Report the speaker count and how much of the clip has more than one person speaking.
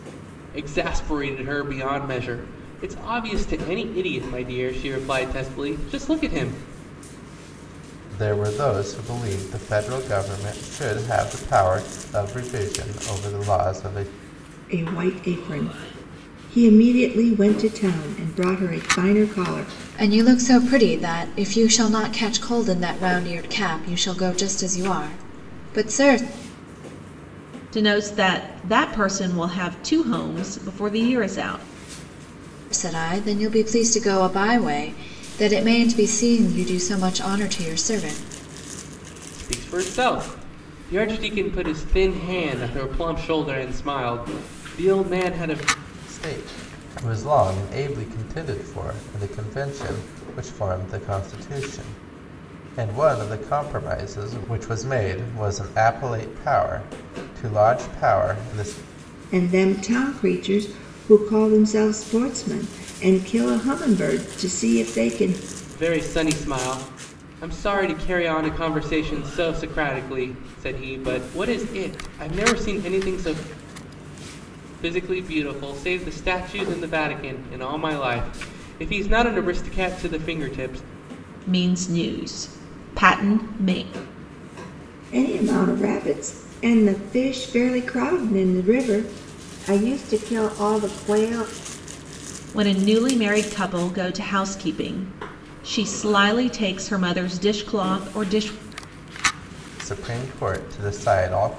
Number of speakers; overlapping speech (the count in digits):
5, no overlap